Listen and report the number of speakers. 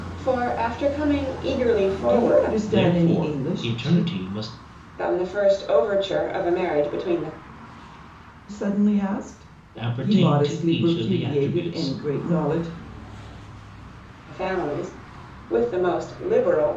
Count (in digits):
3